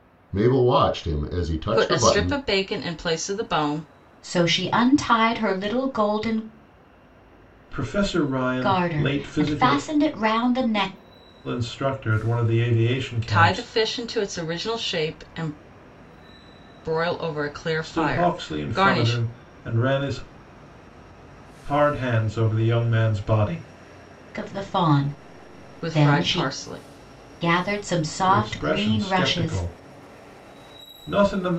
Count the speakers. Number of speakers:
four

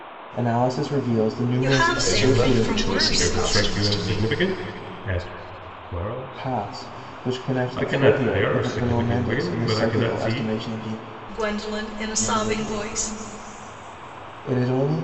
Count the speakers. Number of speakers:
four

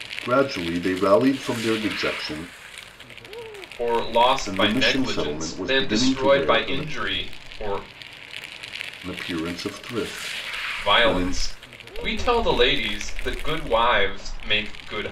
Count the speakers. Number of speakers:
two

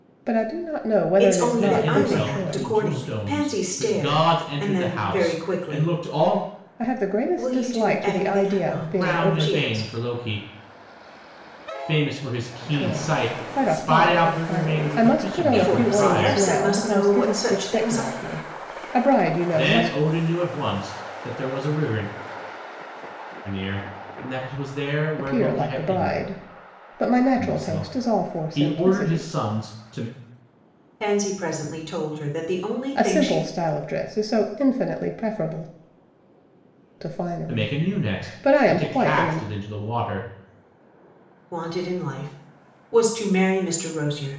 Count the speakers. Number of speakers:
three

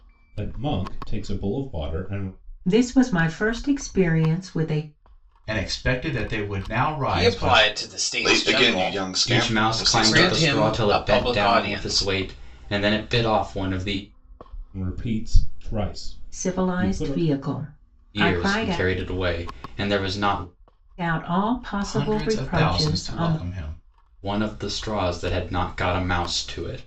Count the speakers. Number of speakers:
six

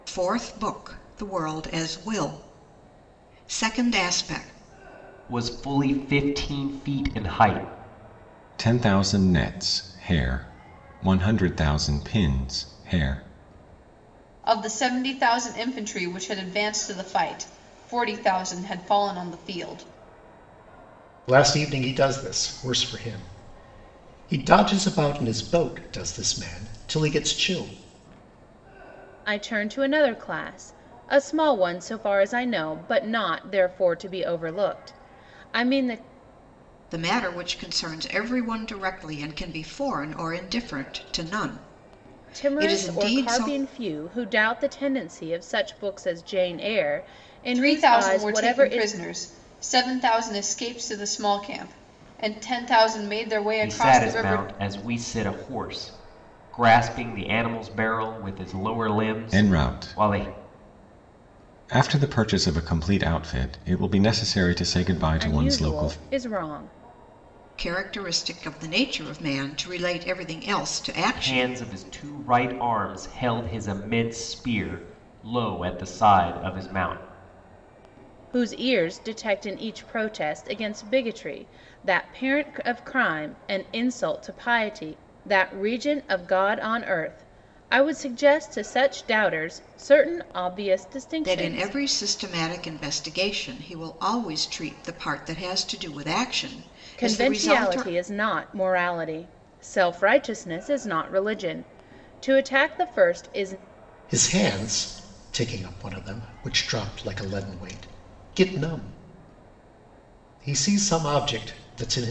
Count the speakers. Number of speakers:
six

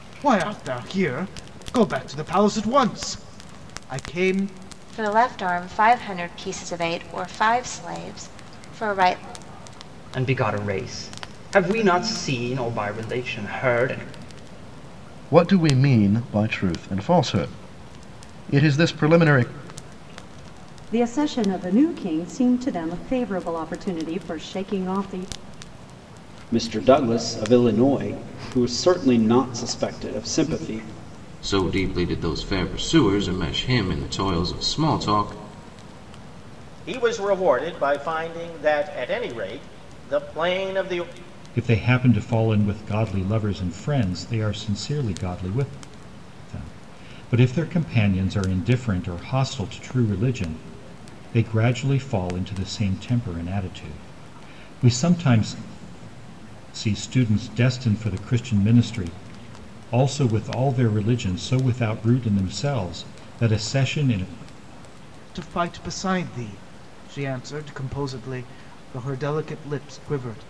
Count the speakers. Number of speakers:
nine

